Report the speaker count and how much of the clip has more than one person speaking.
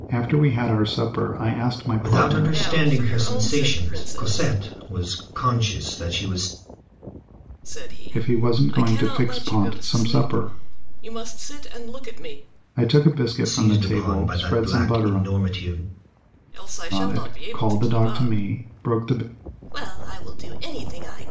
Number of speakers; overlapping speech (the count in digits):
3, about 39%